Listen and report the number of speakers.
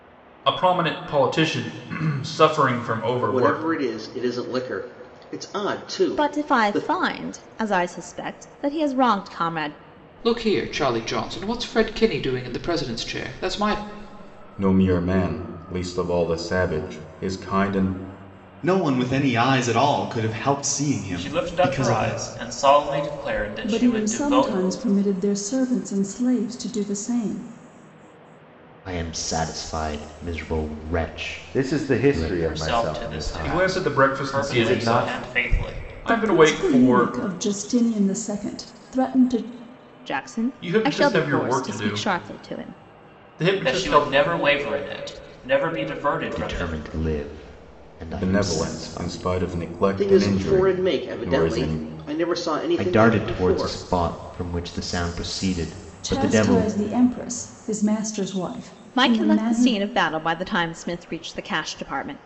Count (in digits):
10